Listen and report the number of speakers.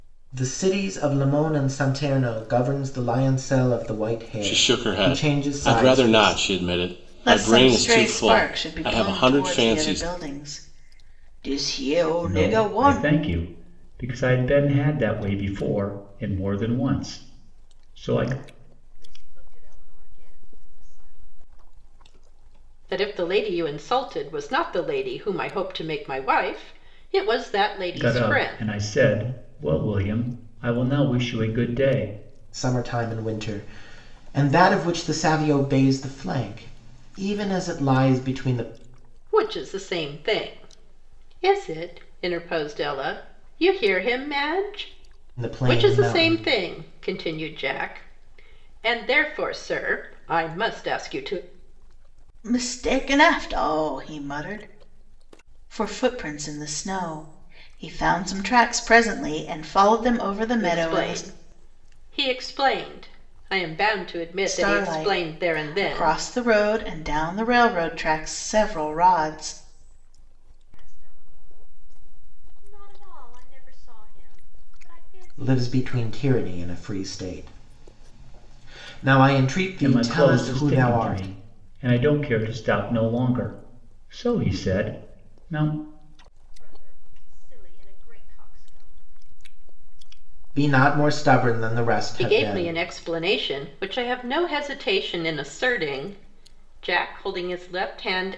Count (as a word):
six